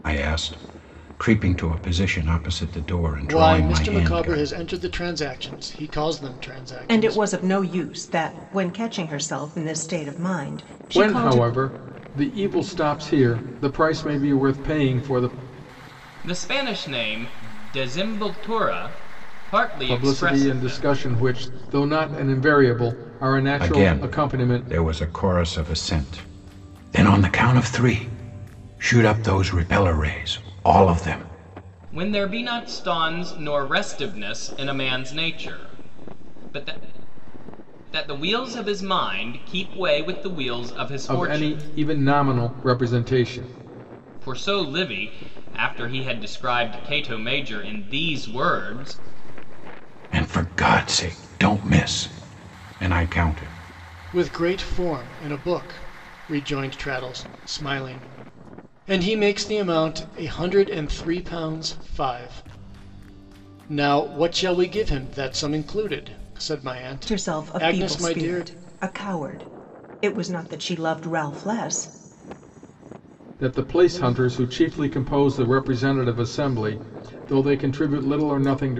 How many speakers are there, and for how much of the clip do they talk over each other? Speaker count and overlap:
5, about 8%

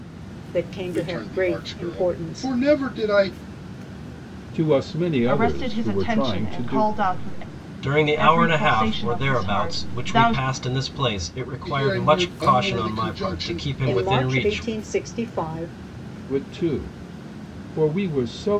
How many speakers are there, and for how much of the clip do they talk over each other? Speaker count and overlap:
5, about 46%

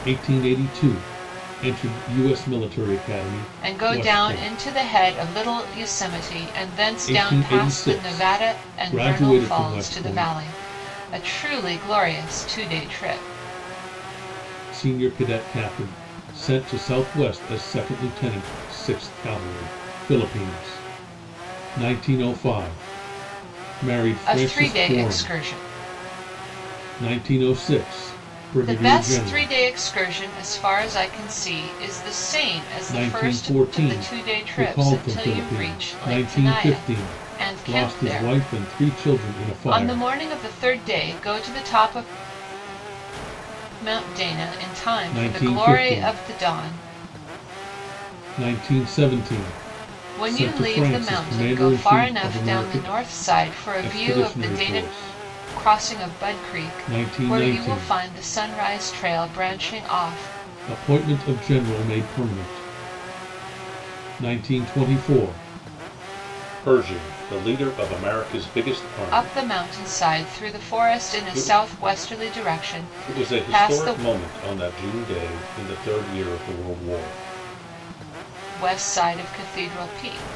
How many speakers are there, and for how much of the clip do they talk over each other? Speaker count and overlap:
2, about 33%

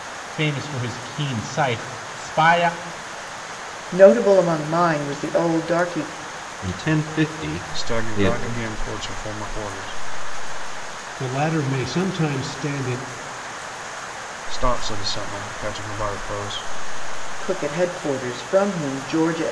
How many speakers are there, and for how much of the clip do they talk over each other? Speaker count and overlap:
5, about 4%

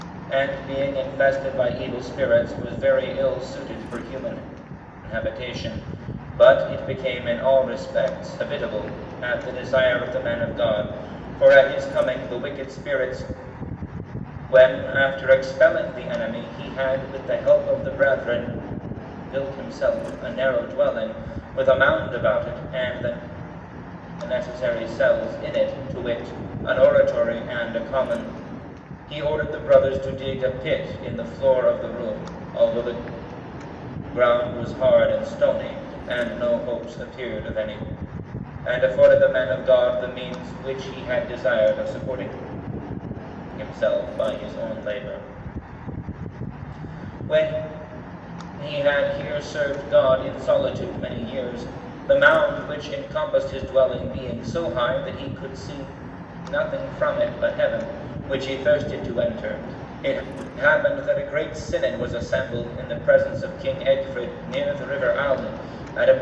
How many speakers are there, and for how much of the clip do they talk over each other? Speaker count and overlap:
1, no overlap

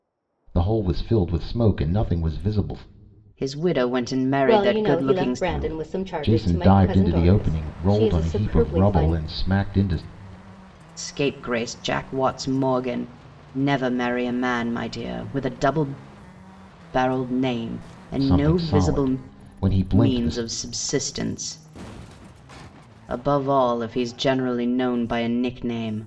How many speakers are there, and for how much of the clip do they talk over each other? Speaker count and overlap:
3, about 24%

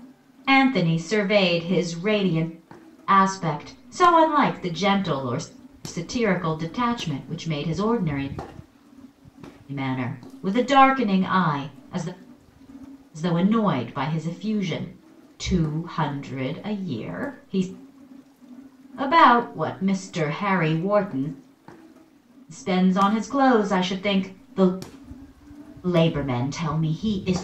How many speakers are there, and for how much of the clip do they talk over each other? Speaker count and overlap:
1, no overlap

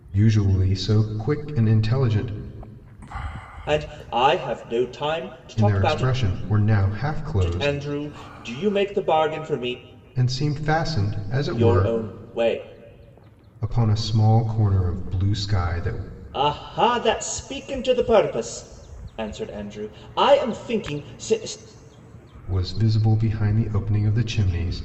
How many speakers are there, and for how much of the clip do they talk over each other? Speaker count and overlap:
2, about 6%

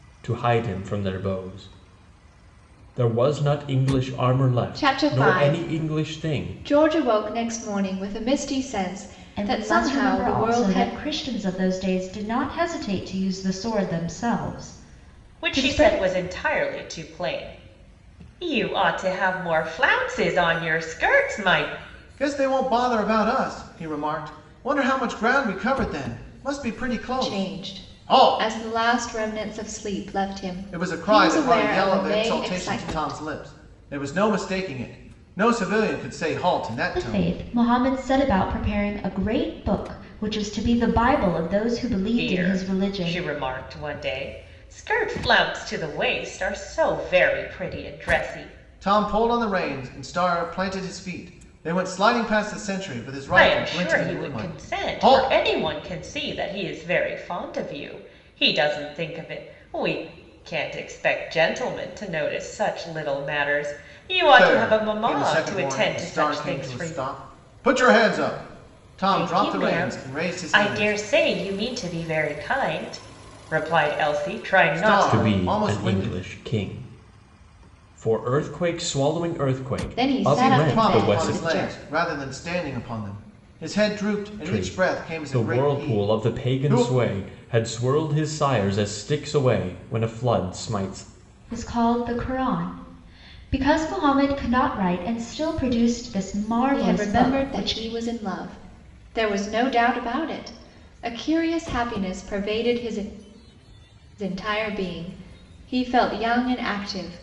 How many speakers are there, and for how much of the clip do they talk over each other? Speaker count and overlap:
5, about 22%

